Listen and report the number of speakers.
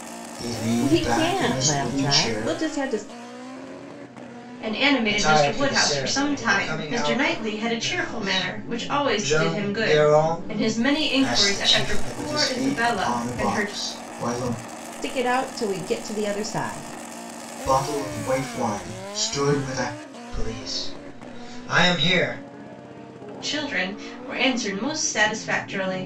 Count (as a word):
four